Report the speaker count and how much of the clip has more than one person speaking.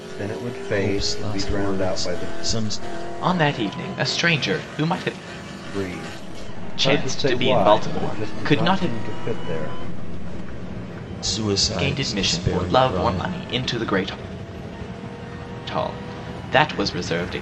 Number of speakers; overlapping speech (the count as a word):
three, about 32%